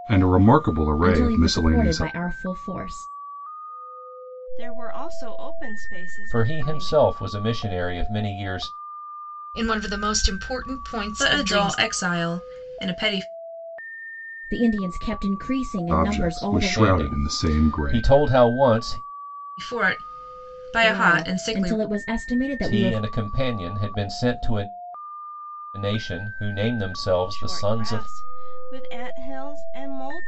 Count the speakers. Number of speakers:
6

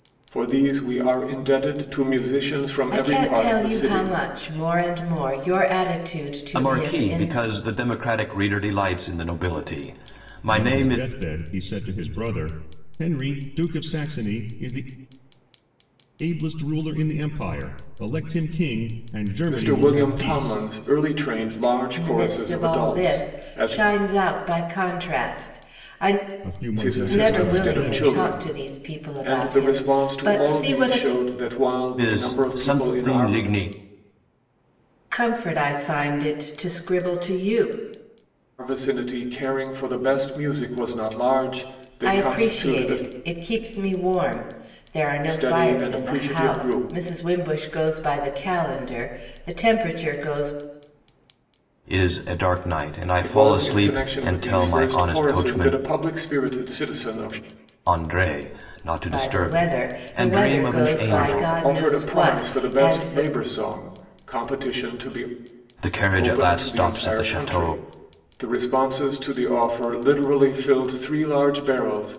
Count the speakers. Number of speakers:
4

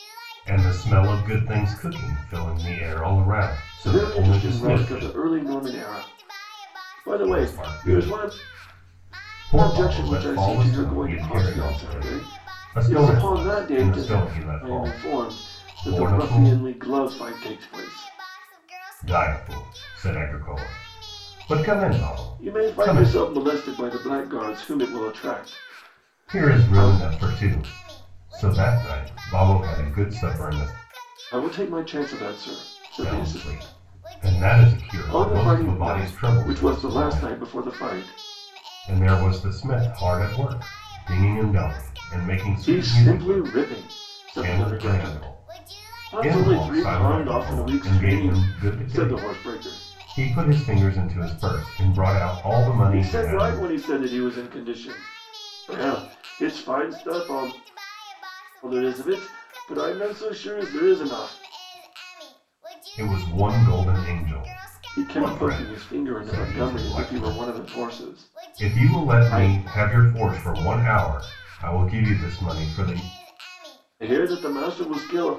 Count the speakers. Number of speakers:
2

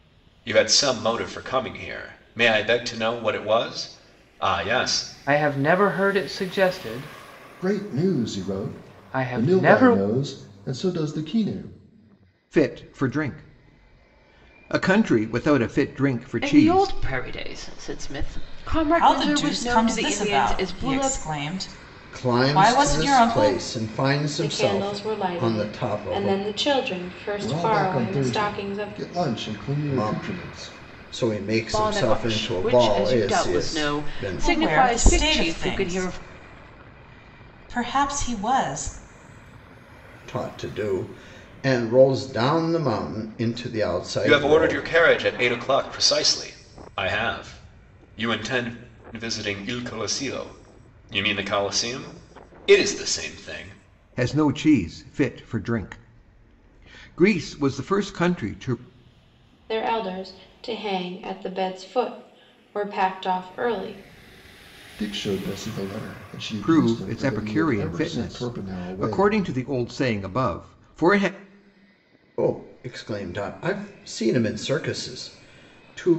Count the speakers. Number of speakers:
8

